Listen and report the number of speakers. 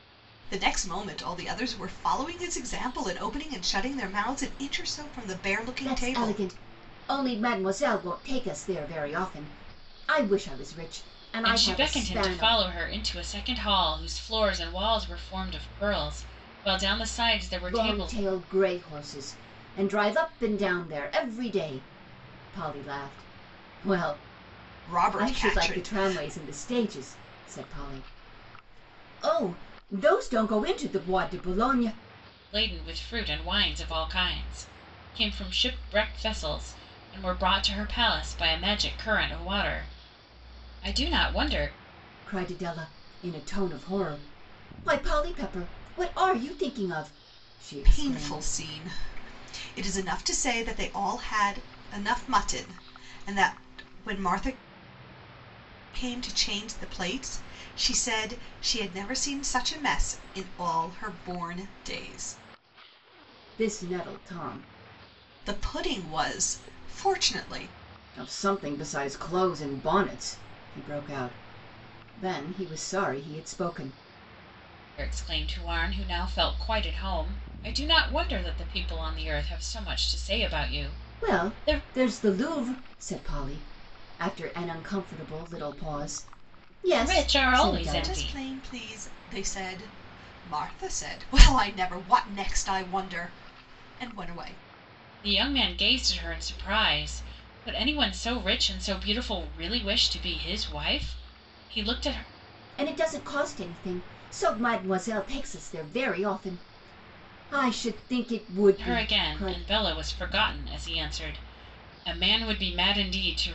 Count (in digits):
3